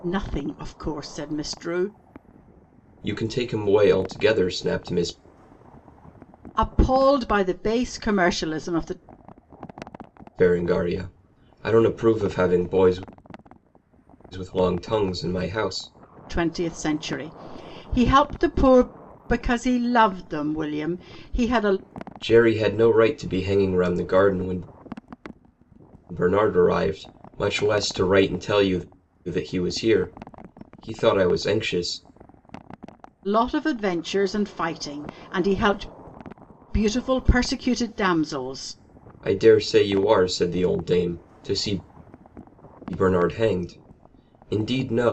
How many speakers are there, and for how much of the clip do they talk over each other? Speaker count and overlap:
2, no overlap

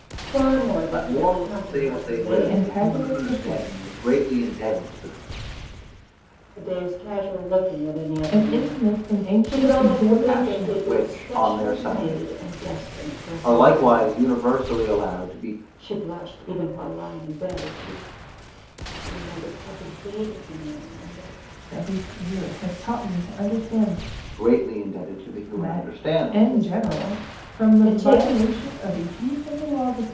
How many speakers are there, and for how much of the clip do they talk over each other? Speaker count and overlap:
3, about 34%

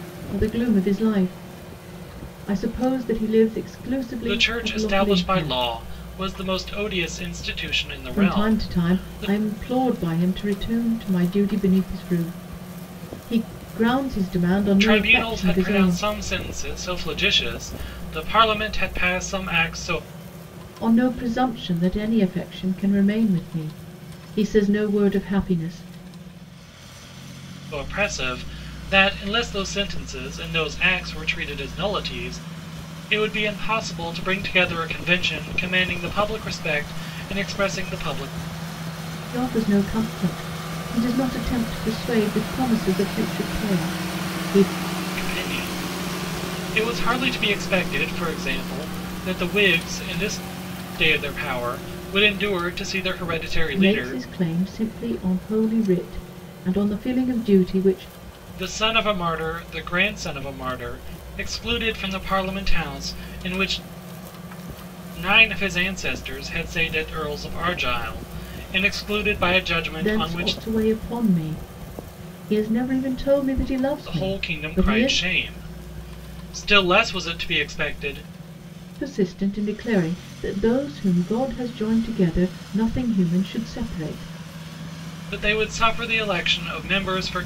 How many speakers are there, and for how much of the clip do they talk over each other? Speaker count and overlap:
2, about 7%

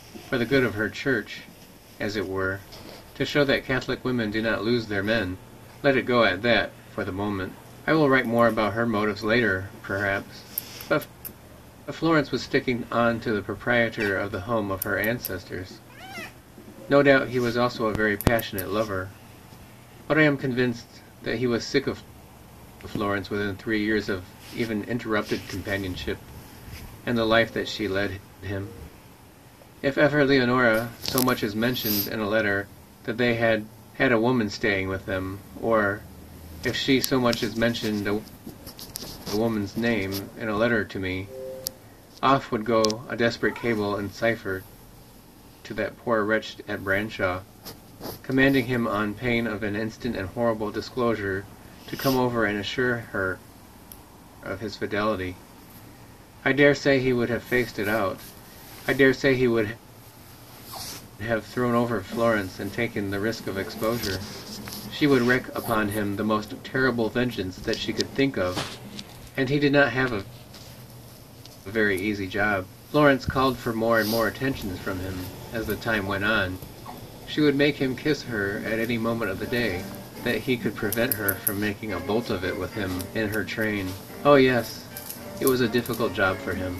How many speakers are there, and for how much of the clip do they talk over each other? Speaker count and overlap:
1, no overlap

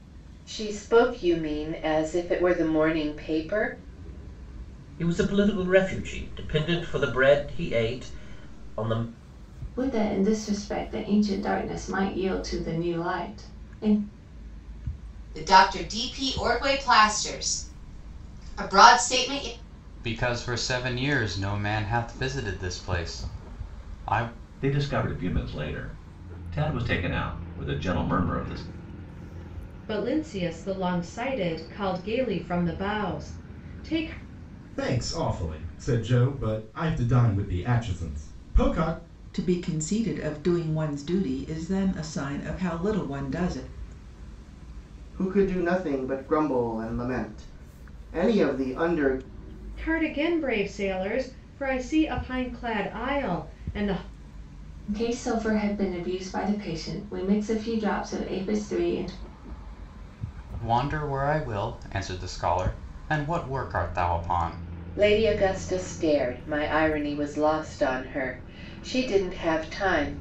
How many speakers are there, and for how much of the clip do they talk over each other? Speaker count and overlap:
10, no overlap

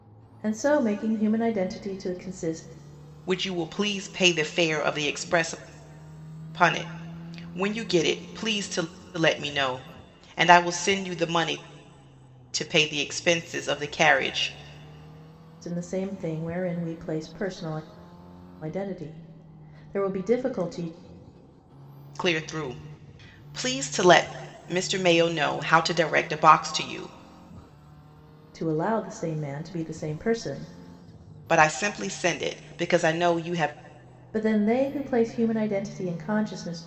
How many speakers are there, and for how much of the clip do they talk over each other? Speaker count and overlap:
2, no overlap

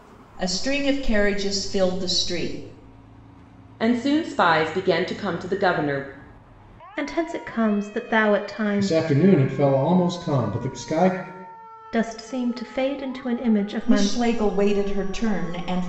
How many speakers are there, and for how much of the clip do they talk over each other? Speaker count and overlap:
4, about 4%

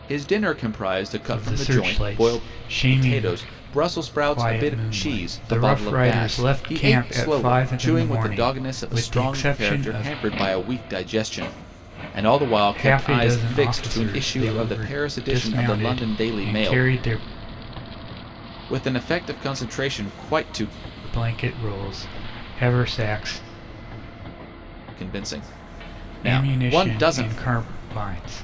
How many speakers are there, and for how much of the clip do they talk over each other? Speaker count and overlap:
2, about 45%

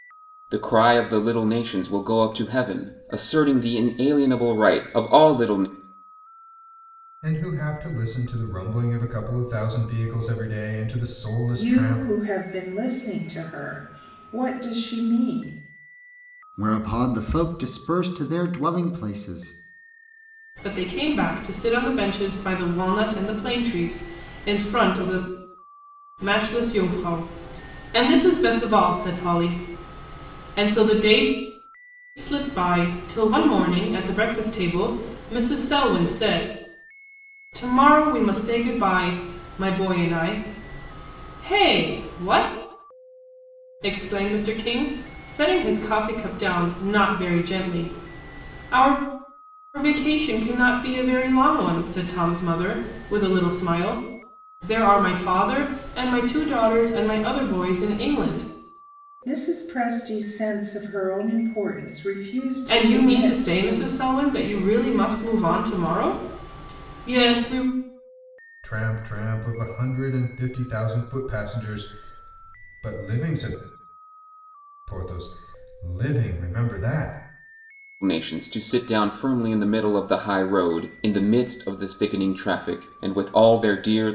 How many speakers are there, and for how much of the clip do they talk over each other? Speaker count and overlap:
5, about 2%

